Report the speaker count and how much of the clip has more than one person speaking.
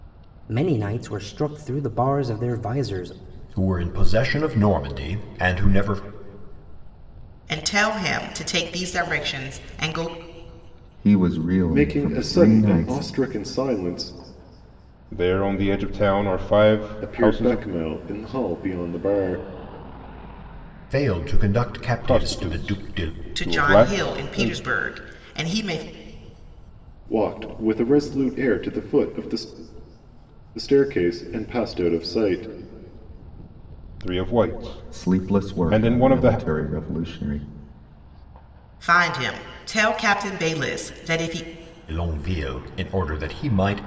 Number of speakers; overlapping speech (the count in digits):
6, about 14%